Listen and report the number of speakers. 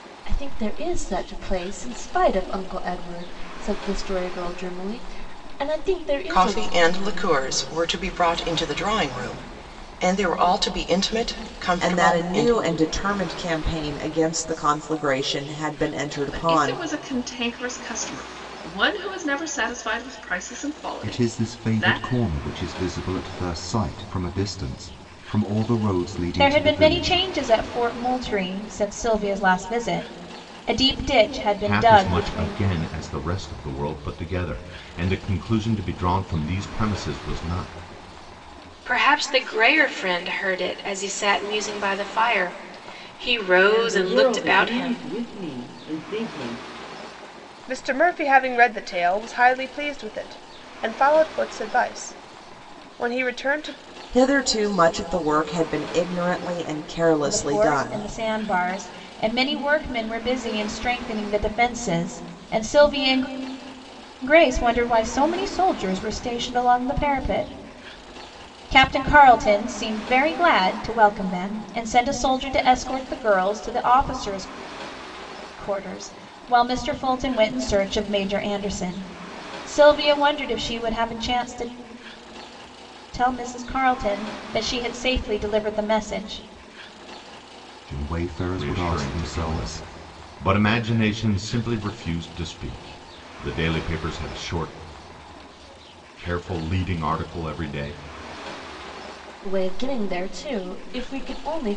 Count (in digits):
10